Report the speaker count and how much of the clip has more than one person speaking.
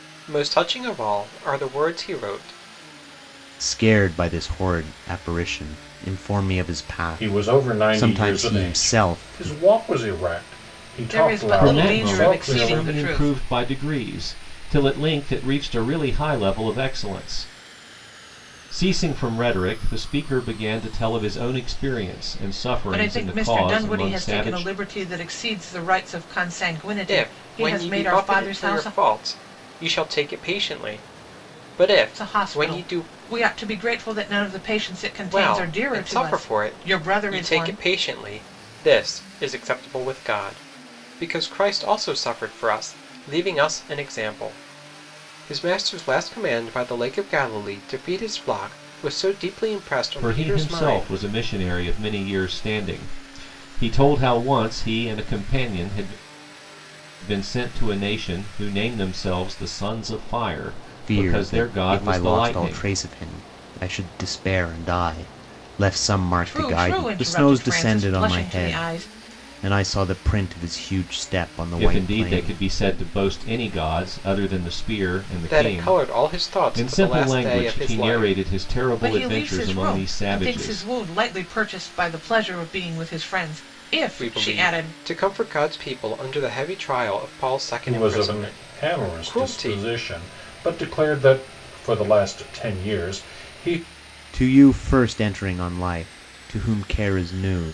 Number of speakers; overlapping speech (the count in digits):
5, about 27%